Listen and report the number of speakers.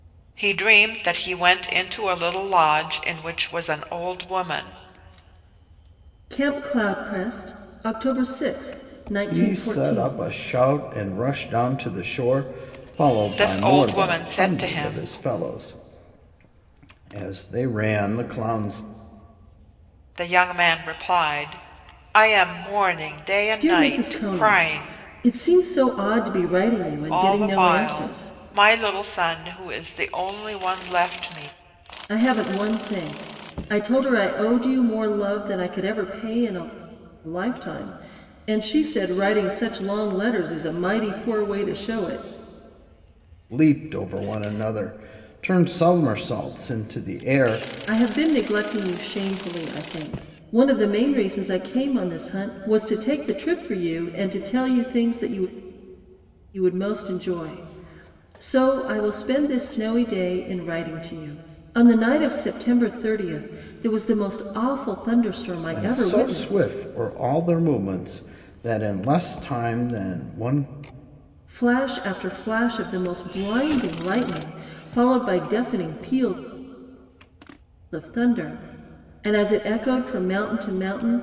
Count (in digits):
3